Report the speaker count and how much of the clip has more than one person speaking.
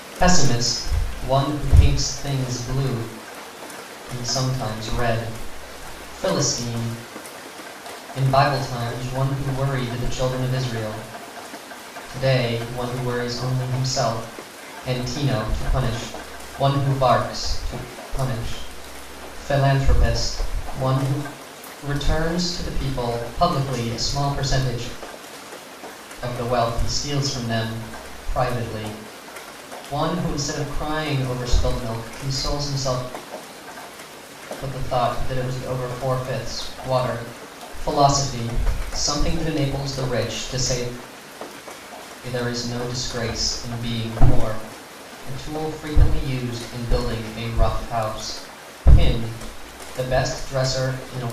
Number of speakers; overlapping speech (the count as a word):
one, no overlap